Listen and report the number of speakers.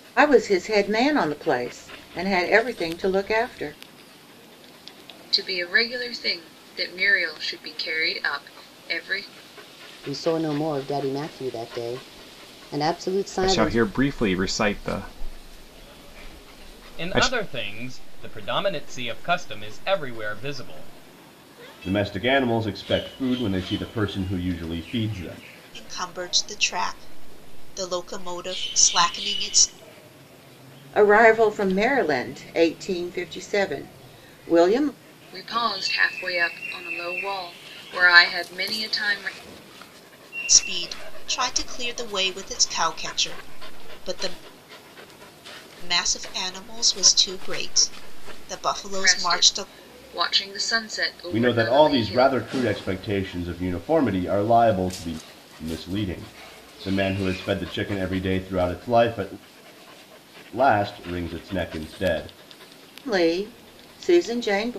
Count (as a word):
seven